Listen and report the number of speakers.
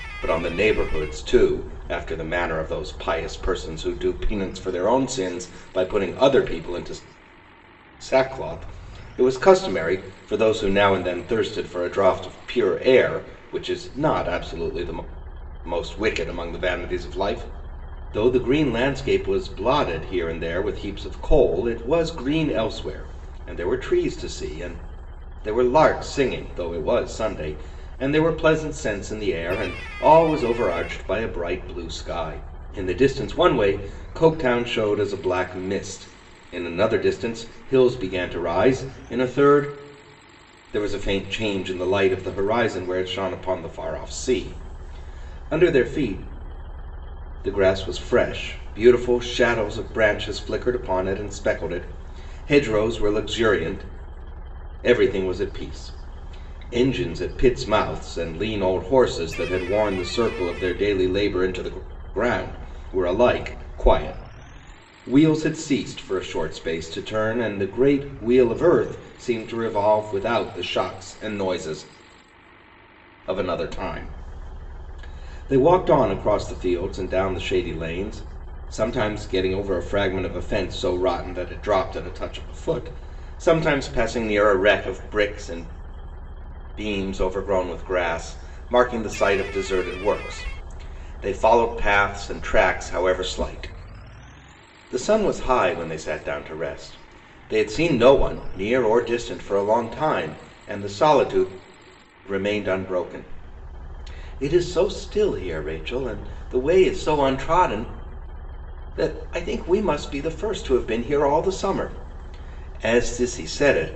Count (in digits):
1